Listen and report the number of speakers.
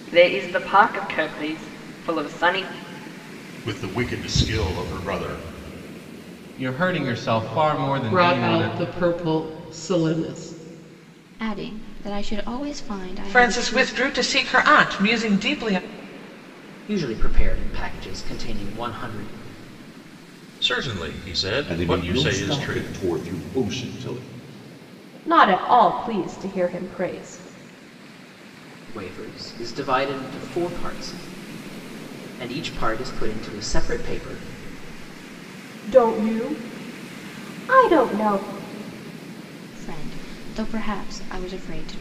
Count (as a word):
ten